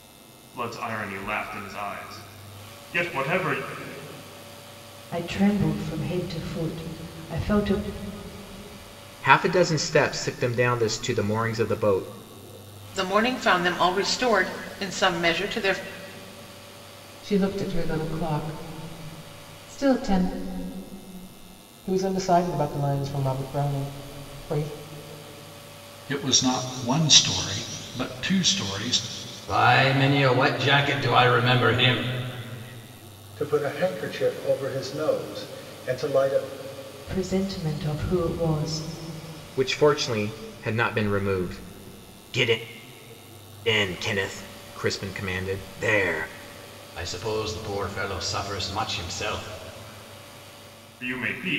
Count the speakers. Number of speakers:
nine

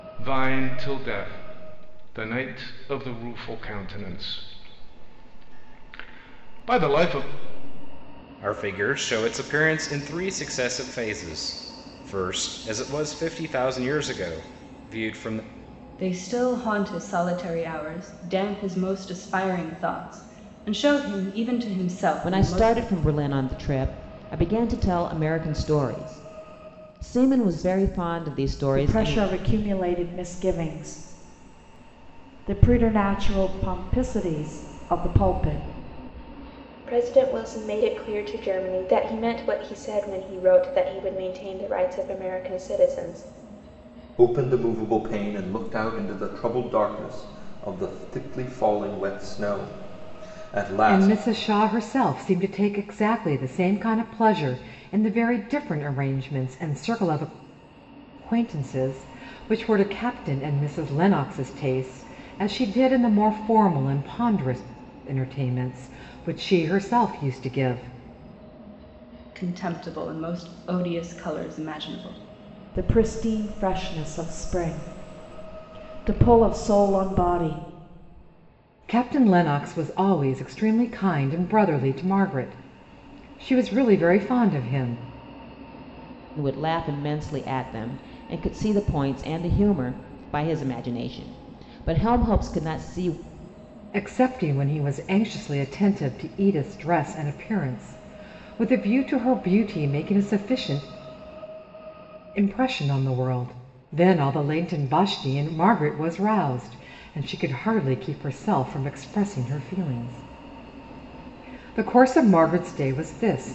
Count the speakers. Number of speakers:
eight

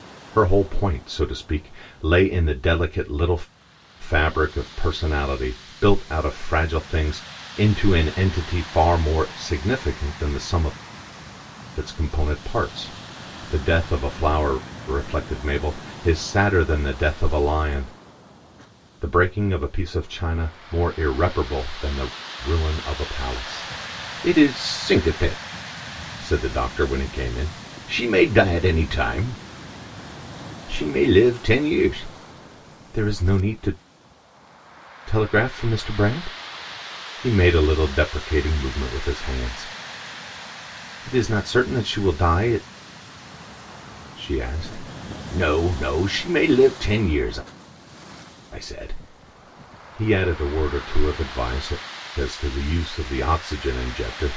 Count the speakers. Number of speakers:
one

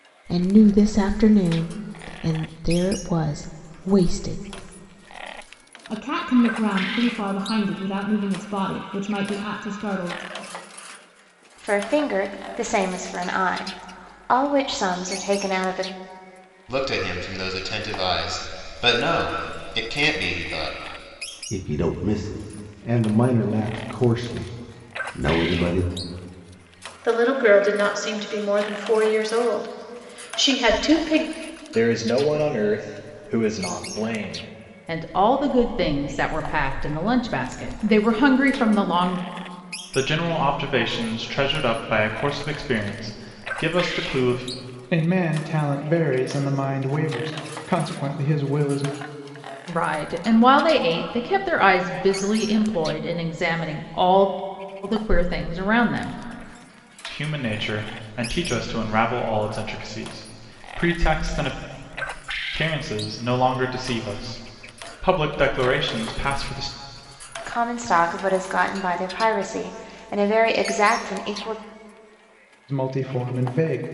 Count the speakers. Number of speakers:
ten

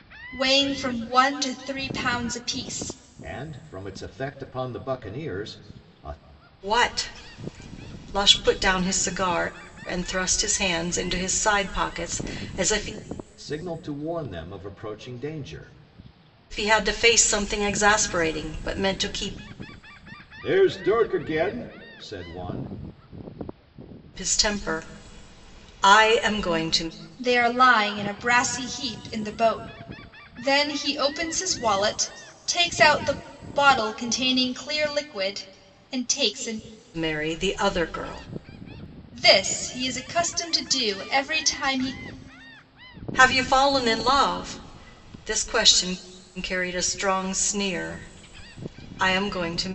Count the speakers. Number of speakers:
three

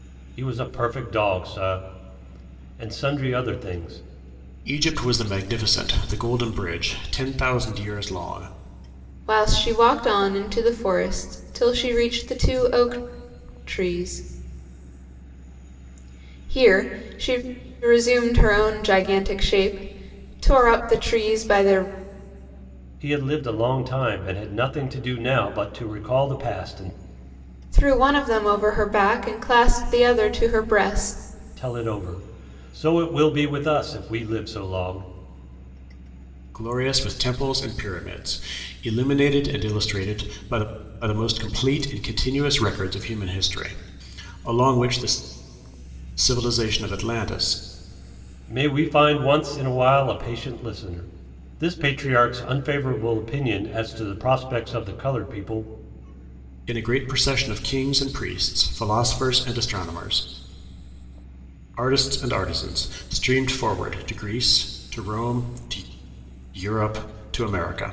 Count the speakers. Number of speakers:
three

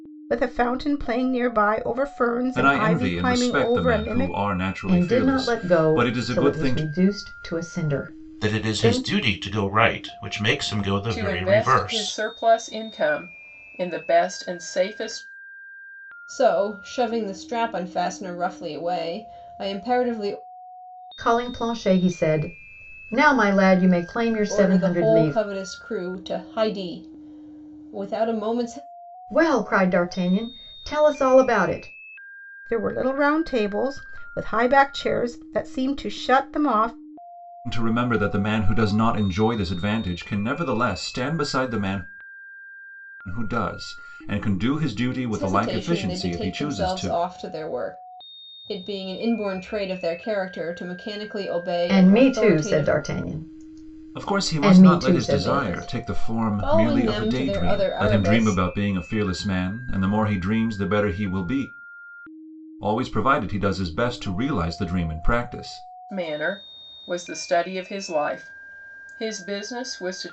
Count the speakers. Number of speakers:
six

